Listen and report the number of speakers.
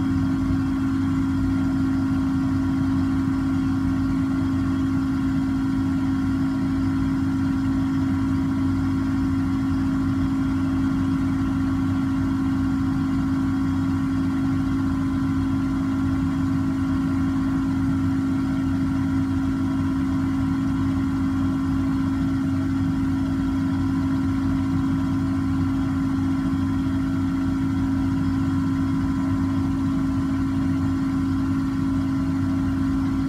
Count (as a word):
zero